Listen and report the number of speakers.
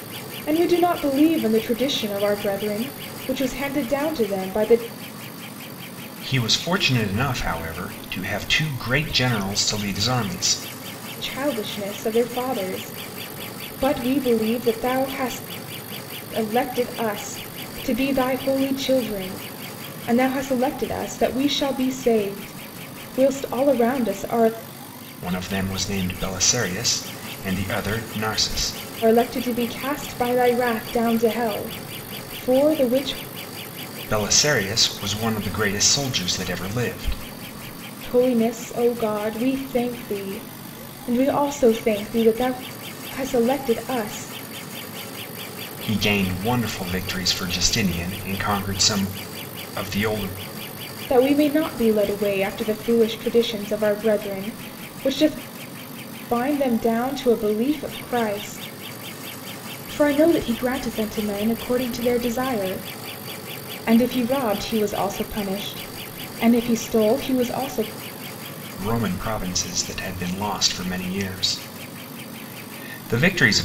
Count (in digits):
2